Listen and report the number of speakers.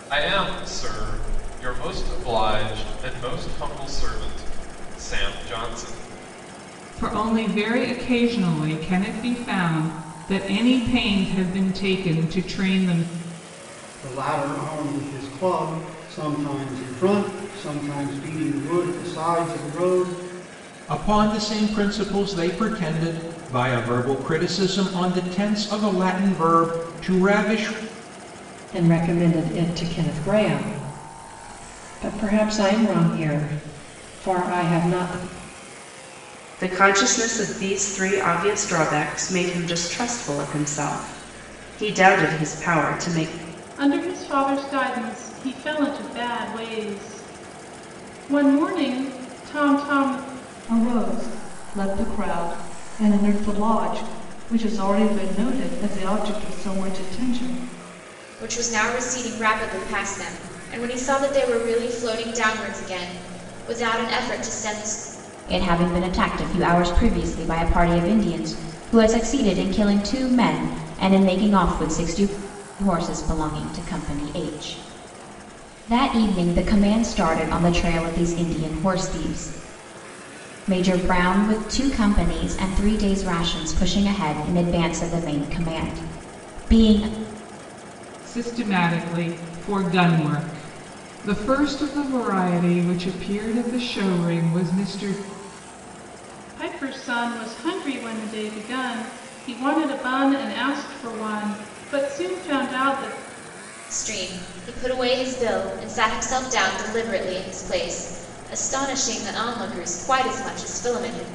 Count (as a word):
ten